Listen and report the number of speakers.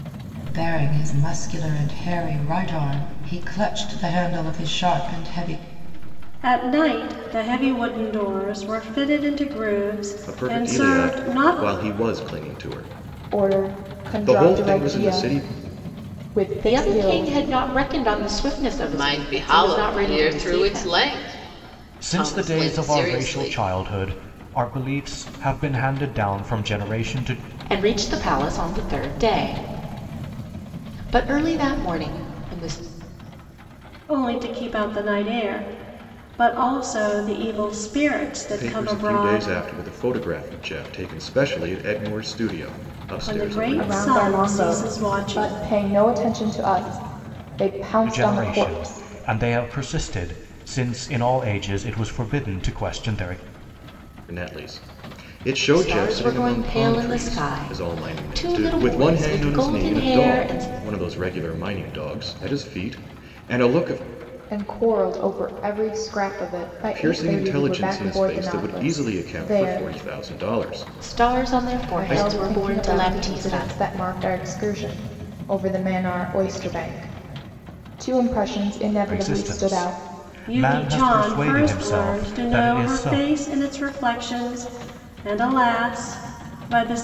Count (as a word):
seven